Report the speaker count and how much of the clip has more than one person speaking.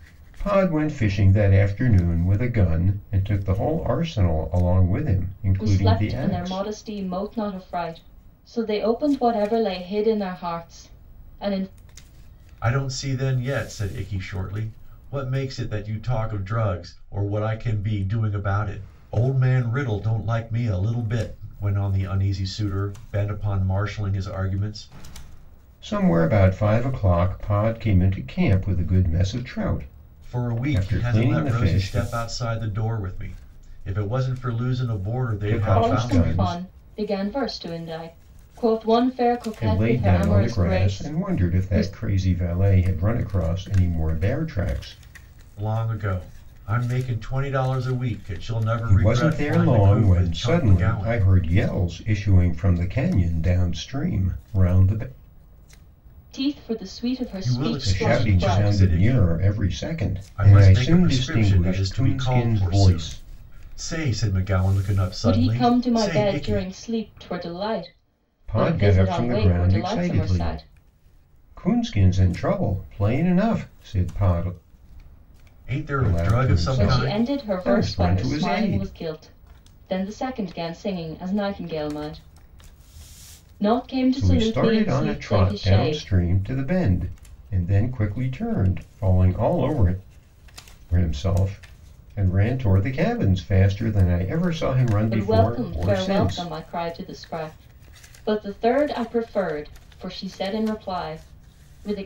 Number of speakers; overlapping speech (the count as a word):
three, about 24%